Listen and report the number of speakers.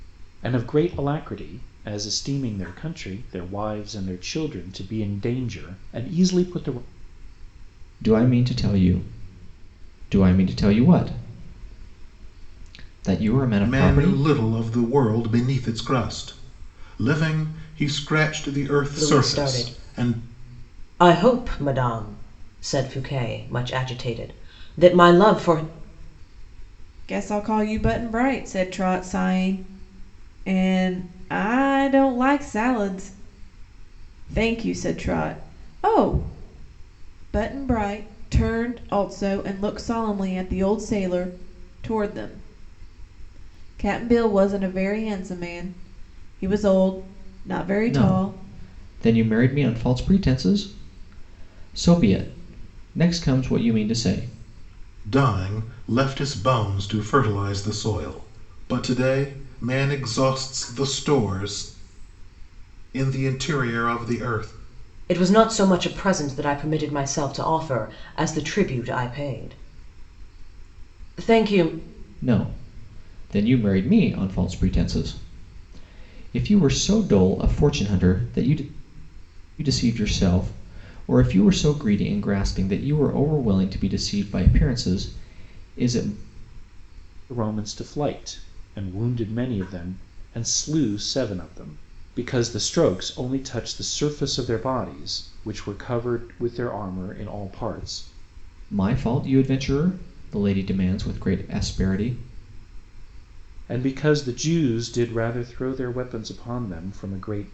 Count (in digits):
5